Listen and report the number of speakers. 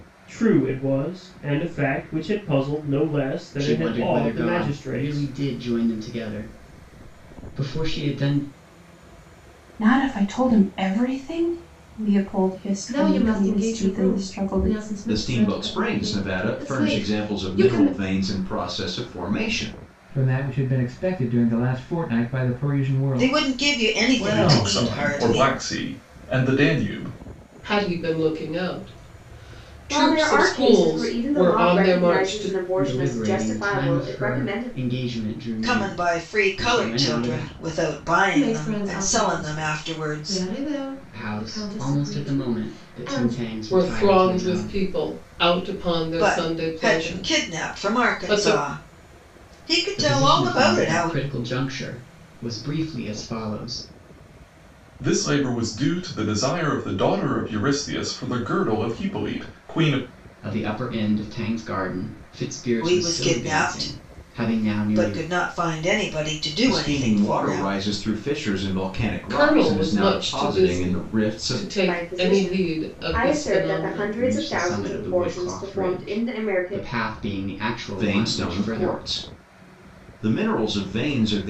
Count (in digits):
10